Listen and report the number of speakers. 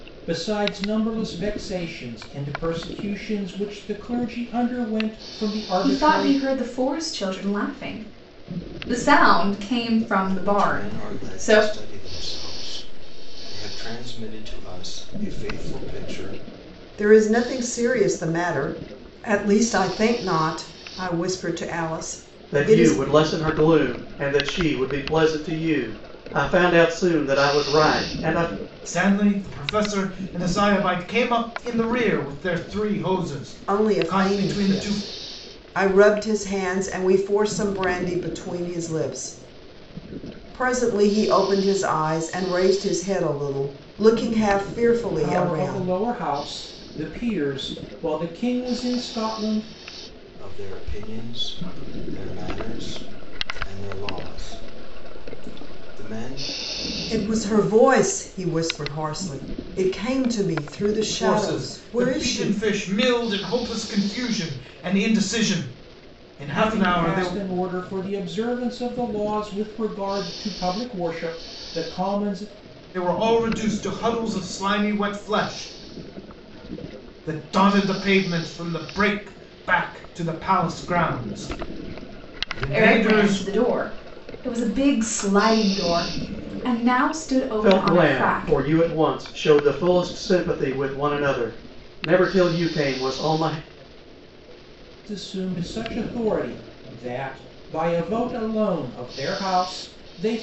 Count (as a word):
six